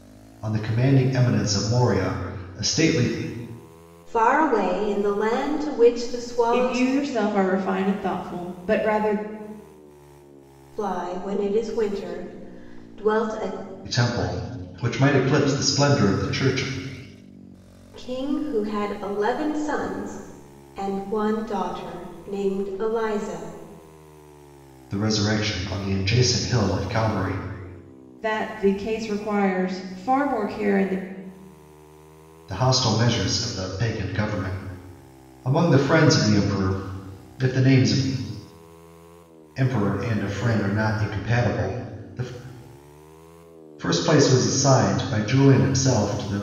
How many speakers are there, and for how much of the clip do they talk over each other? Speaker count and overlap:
3, about 1%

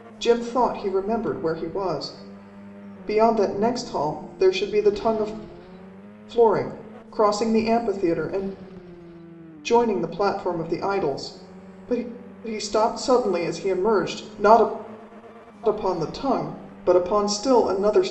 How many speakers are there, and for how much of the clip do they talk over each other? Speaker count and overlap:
1, no overlap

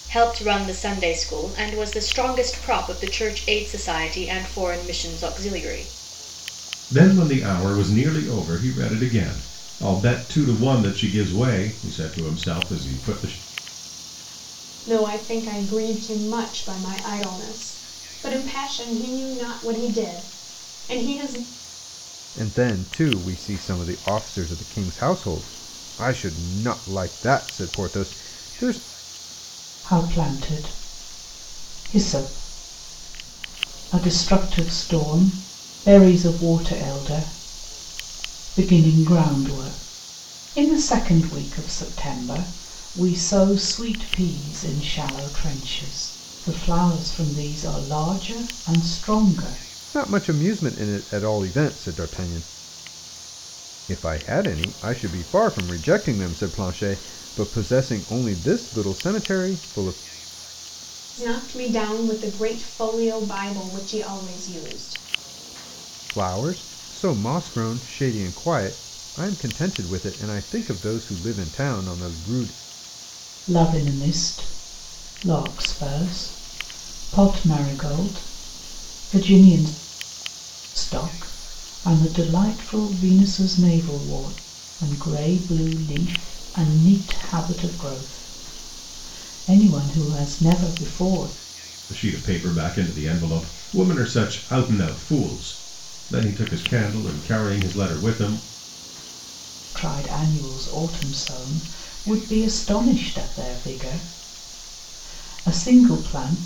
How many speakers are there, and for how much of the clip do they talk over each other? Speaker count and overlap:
5, no overlap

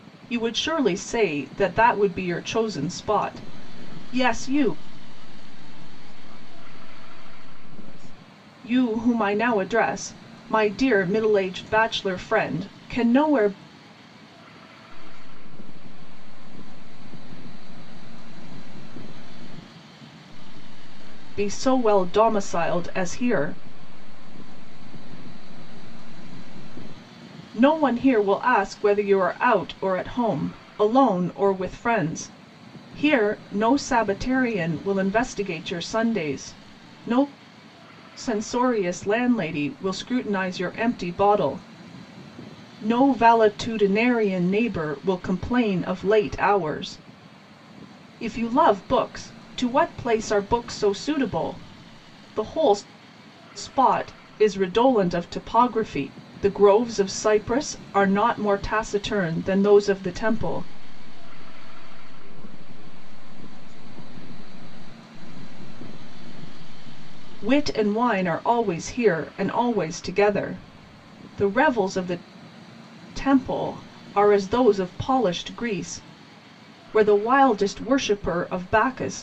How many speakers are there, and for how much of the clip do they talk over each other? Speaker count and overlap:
2, about 5%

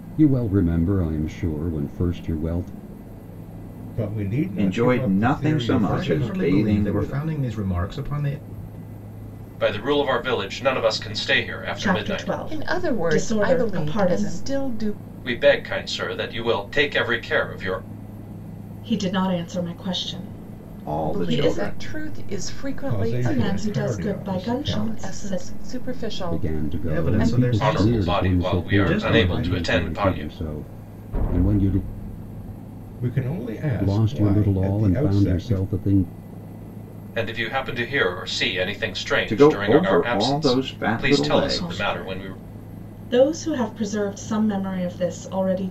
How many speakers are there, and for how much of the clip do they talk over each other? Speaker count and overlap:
7, about 40%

